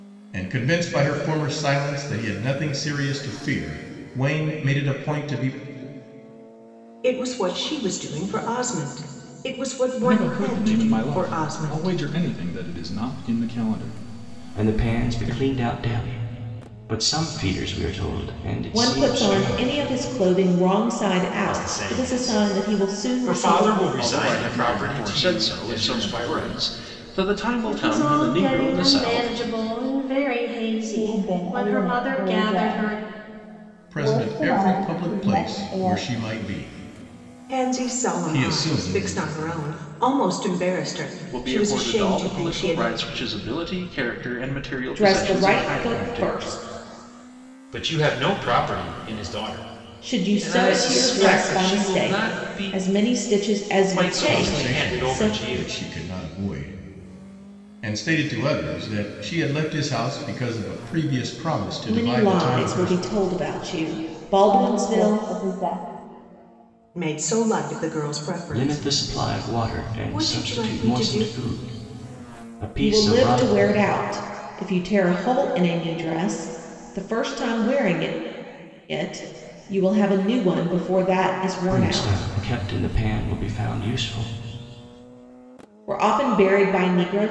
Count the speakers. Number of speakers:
9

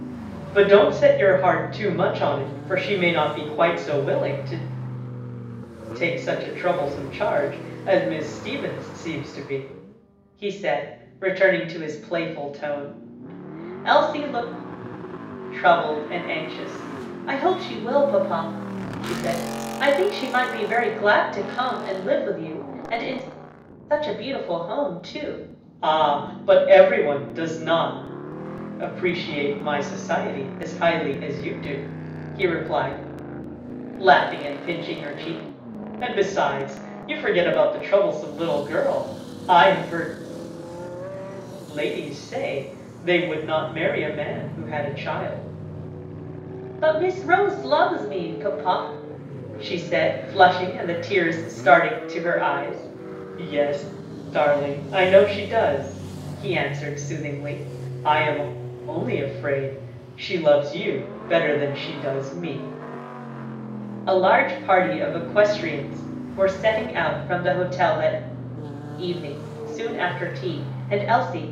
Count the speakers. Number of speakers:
1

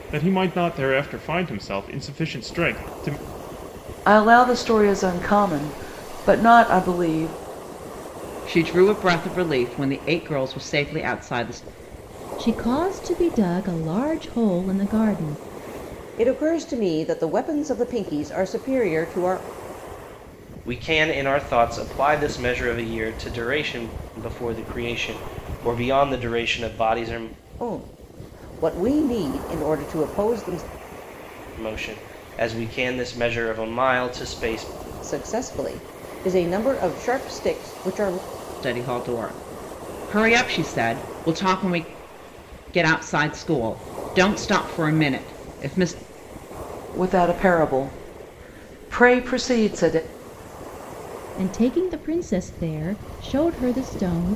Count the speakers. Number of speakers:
6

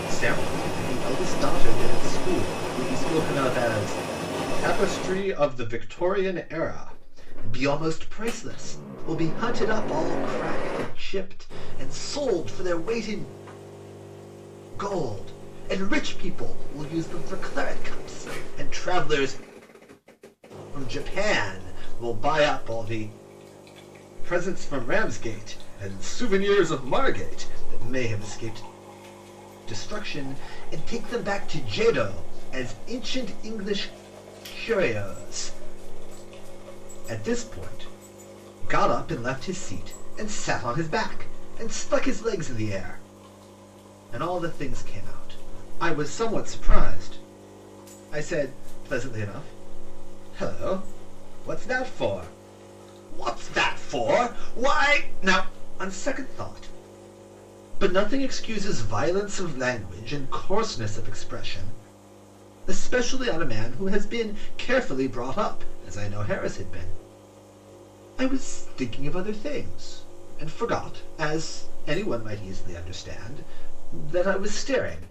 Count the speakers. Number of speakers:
1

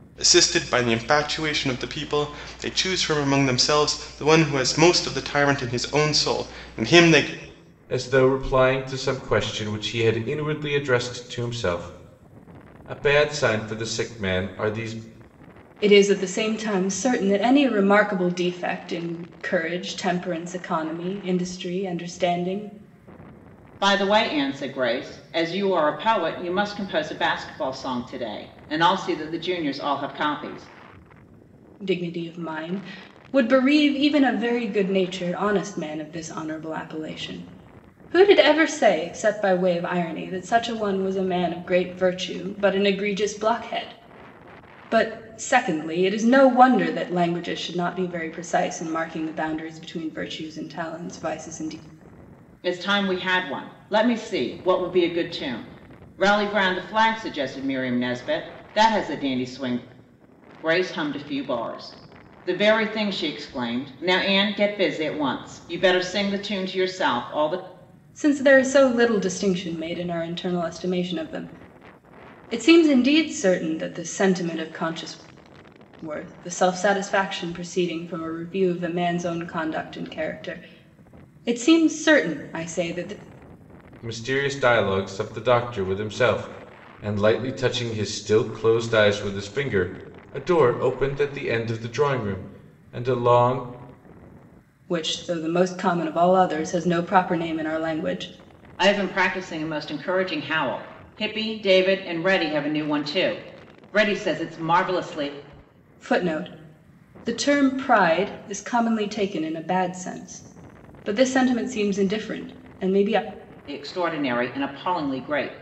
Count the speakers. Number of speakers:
4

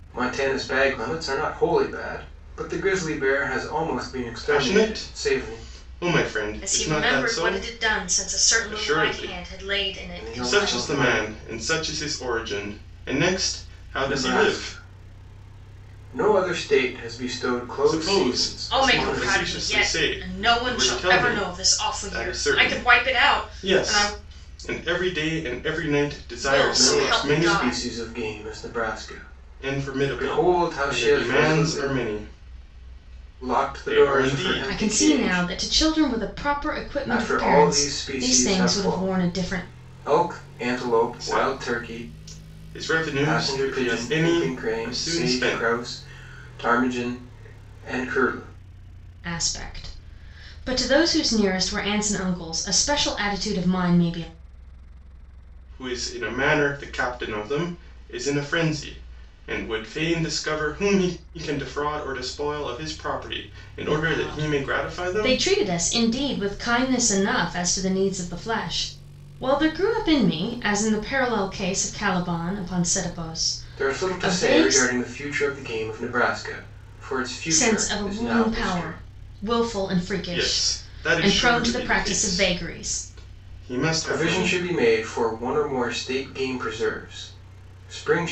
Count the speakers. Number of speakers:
3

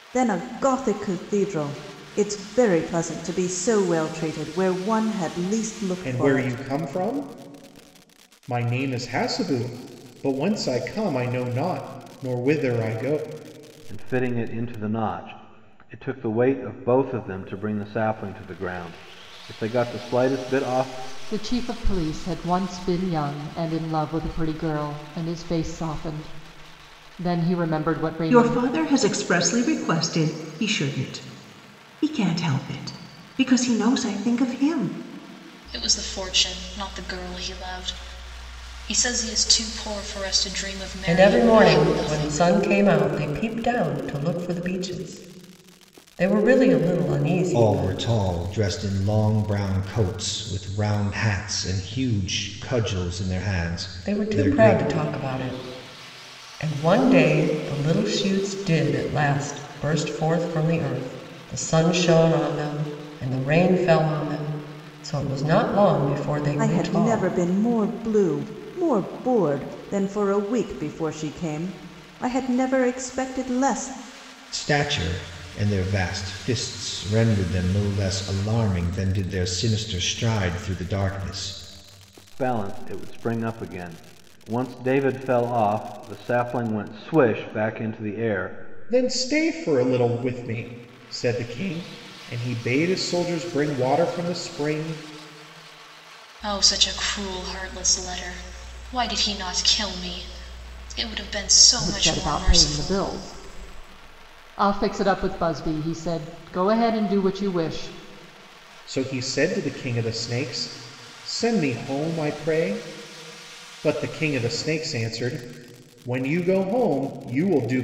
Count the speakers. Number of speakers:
8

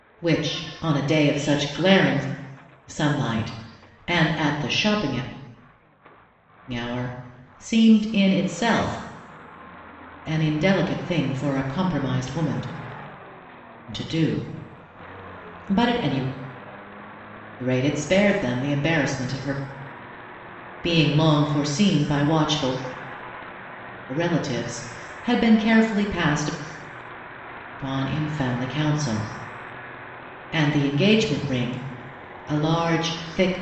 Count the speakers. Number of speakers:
1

